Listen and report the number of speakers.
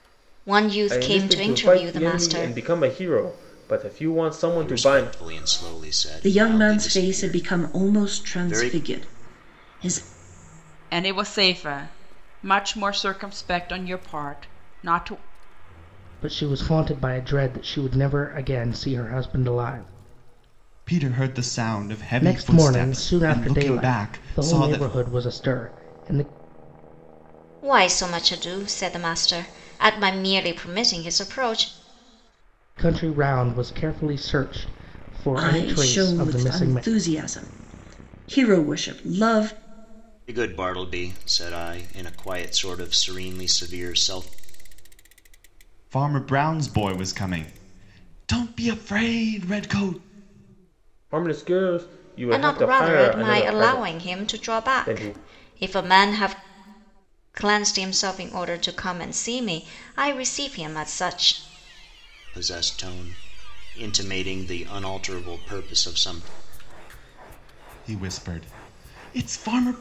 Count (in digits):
7